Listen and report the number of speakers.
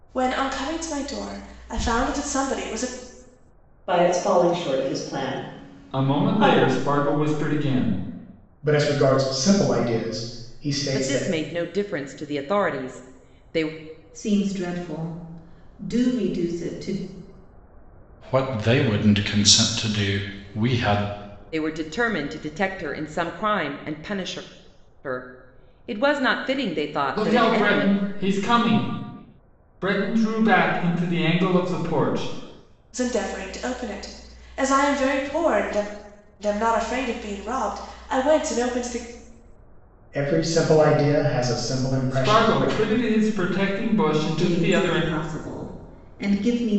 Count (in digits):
7